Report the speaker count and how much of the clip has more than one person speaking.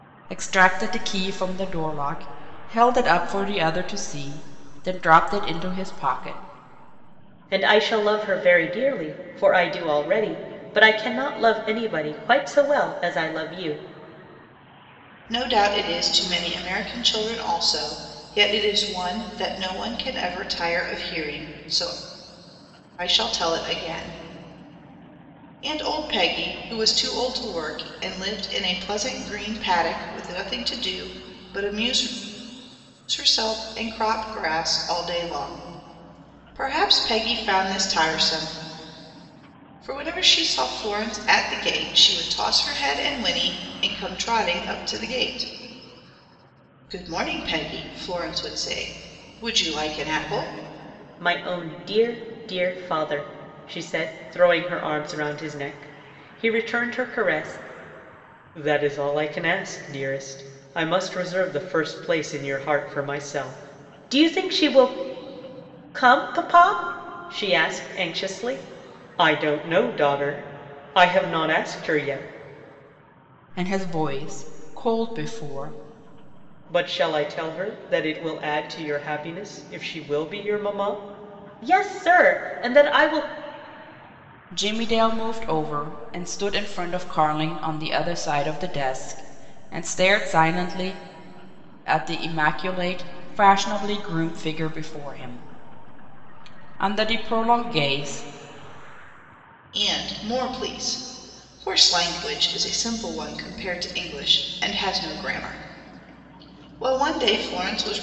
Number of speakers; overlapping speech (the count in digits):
3, no overlap